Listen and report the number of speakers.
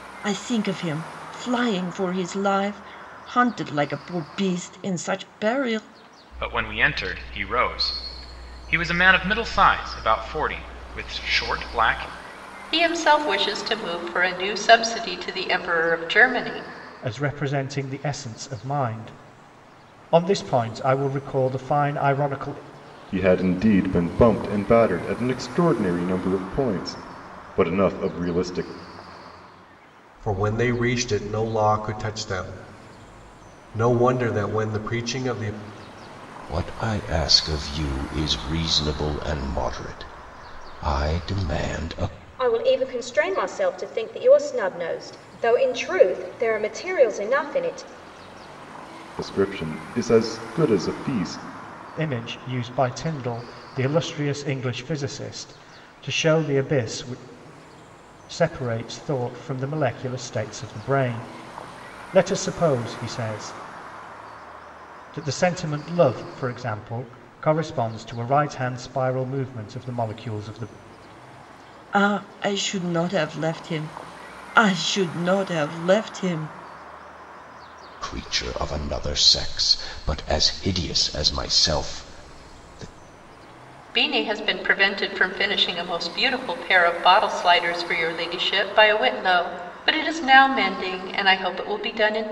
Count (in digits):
8